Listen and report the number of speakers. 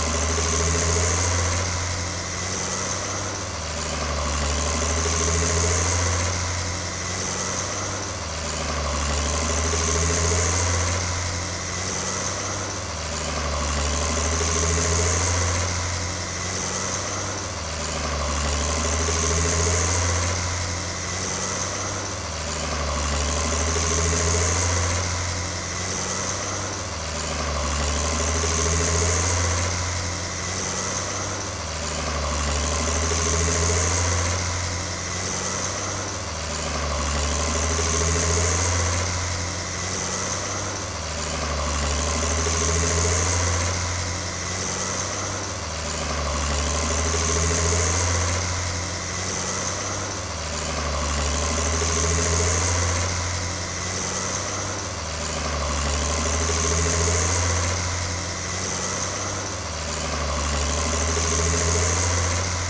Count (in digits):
0